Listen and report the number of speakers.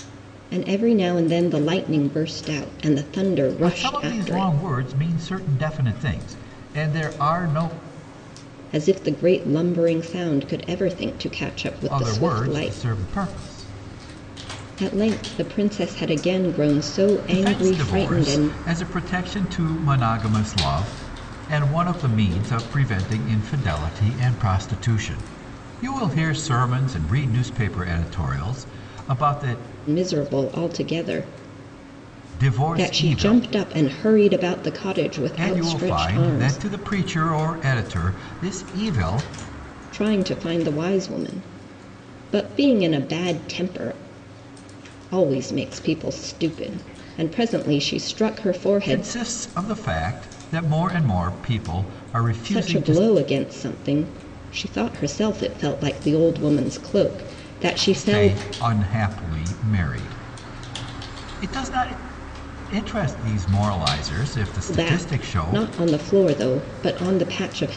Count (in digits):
2